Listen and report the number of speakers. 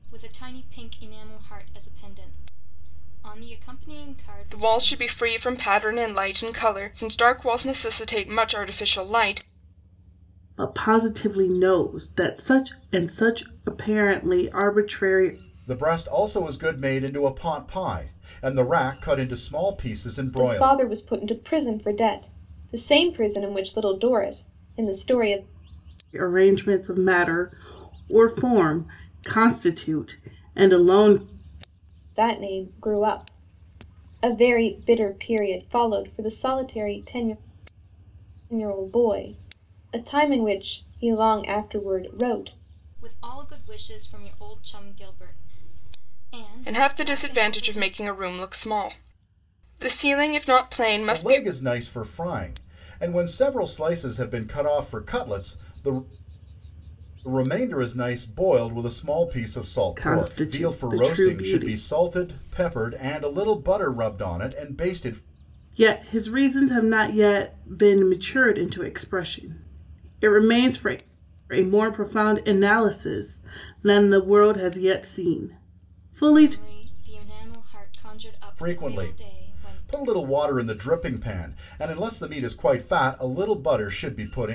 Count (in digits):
5